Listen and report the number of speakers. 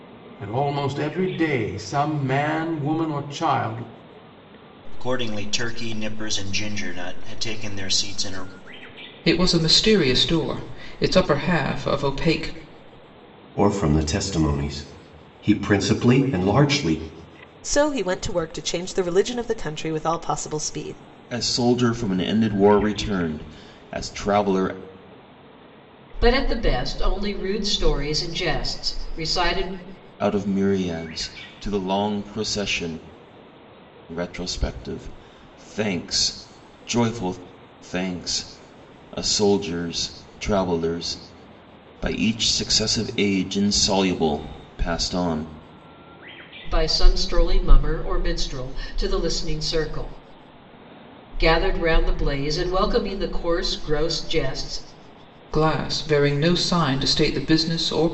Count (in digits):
7